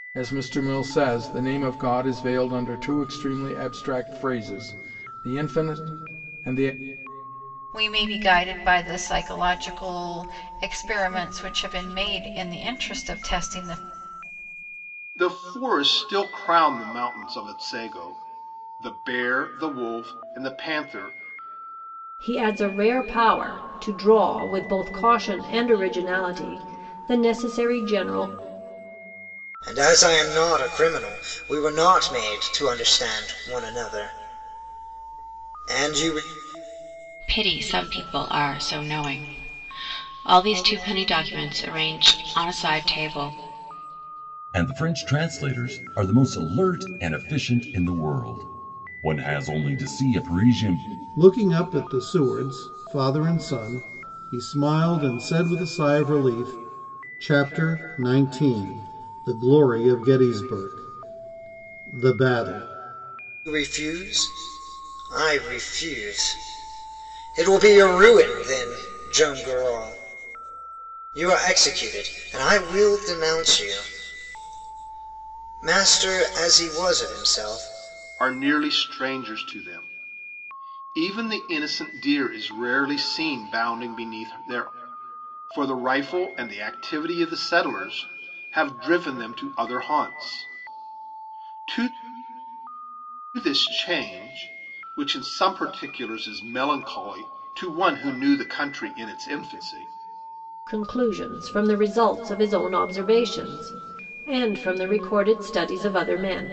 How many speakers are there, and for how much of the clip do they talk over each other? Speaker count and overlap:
eight, no overlap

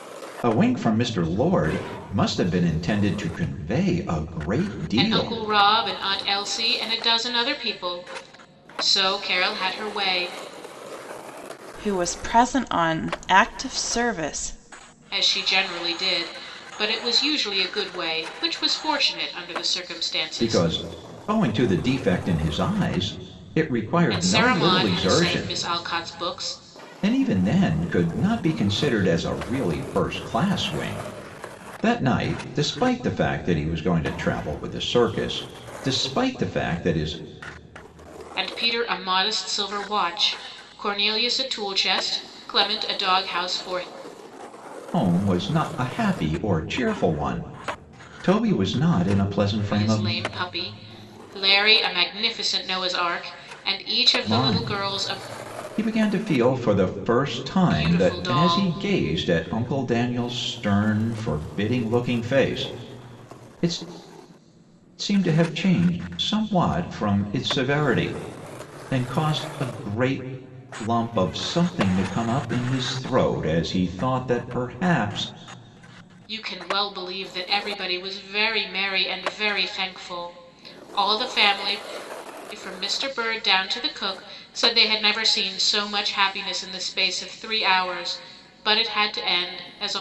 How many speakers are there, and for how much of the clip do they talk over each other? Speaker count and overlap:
three, about 5%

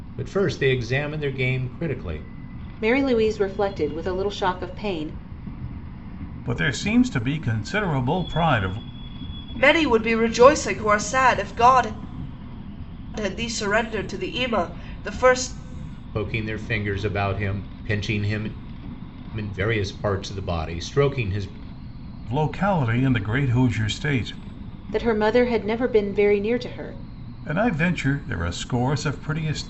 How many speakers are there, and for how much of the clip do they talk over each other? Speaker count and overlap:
four, no overlap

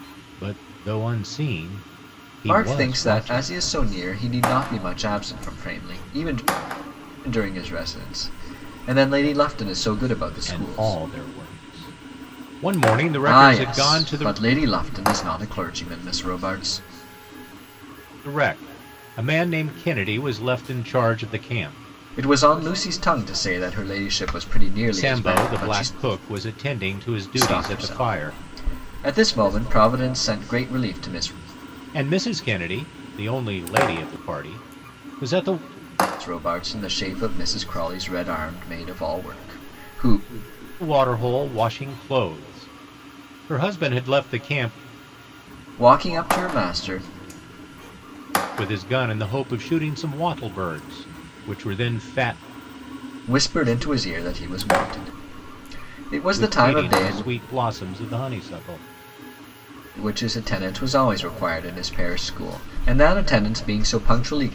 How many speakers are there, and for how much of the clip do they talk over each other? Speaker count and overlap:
two, about 9%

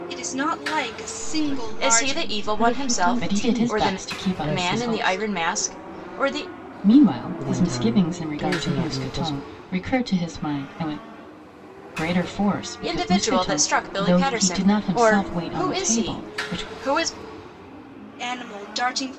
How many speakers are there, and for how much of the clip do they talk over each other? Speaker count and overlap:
five, about 51%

